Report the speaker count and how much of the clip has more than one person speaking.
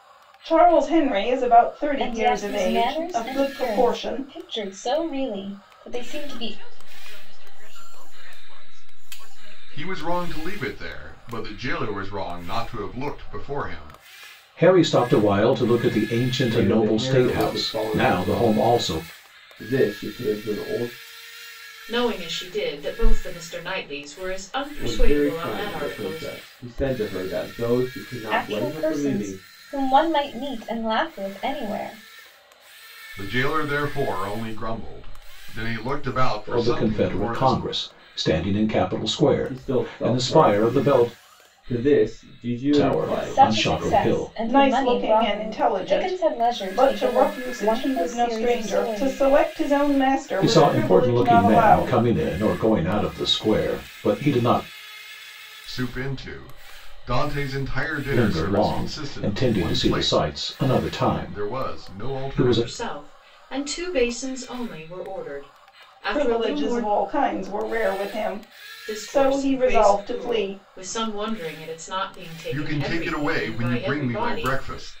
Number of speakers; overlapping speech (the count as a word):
seven, about 38%